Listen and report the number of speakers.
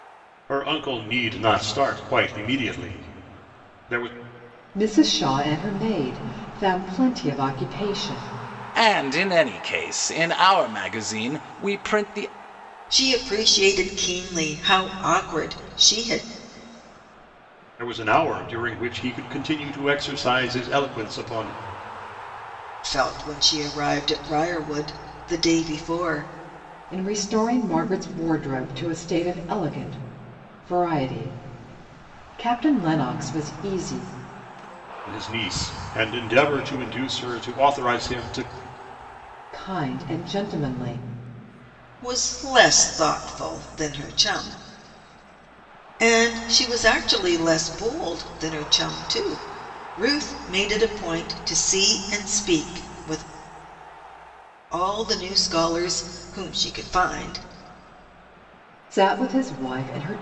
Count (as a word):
four